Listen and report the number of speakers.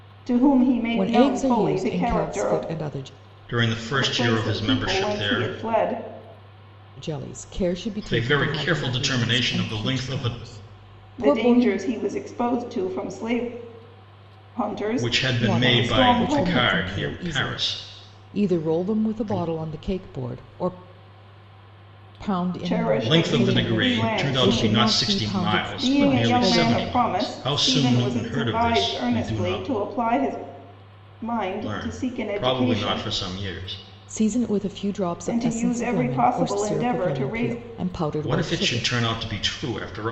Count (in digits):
3